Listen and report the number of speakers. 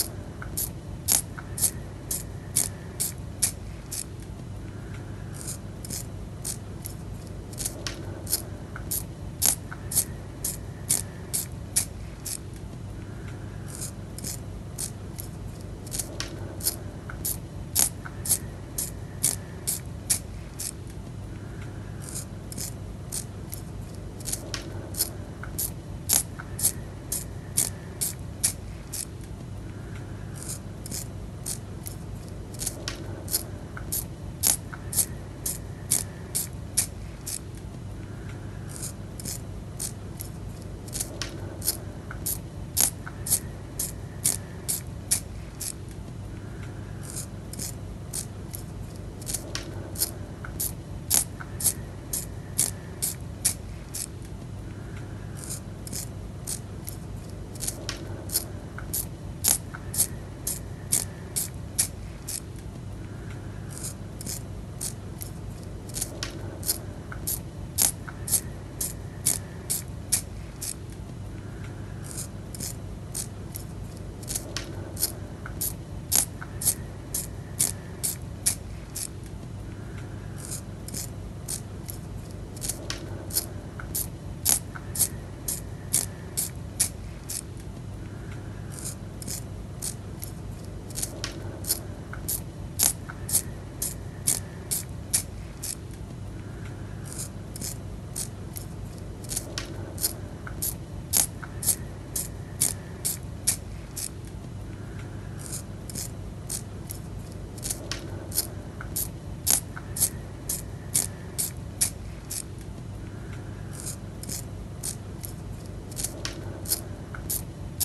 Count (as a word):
zero